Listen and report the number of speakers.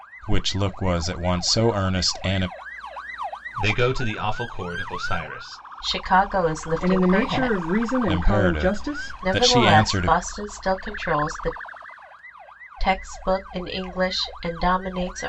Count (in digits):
4